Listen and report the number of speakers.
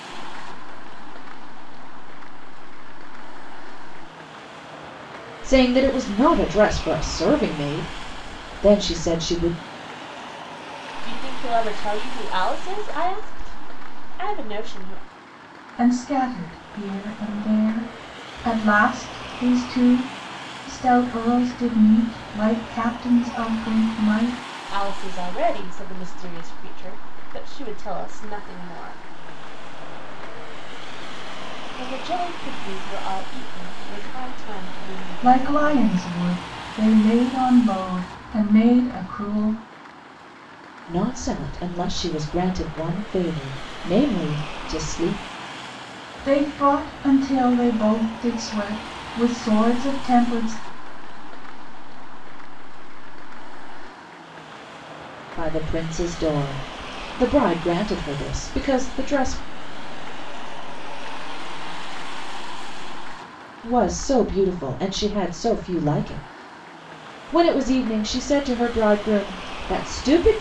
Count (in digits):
4